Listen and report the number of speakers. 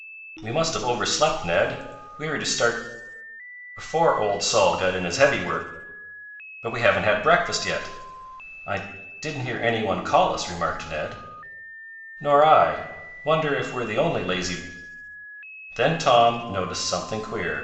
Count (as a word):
one